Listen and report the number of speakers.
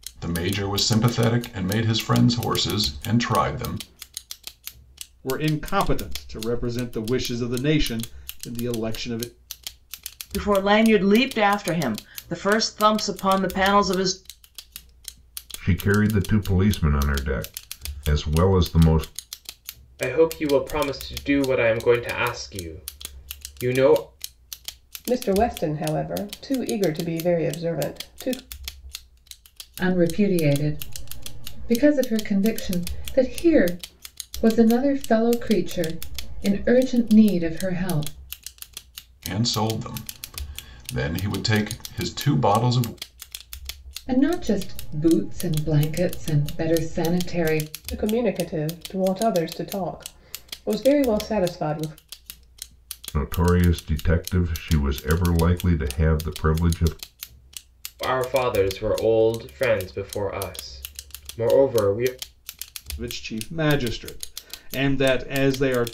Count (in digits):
7